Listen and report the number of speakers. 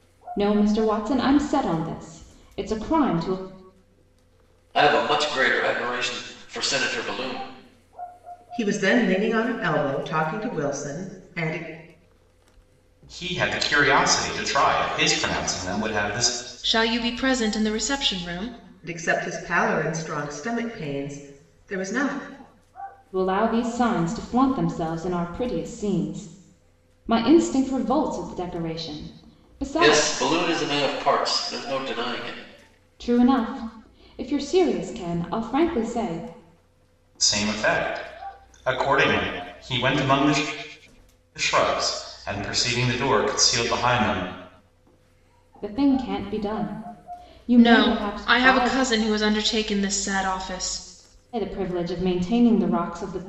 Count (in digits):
5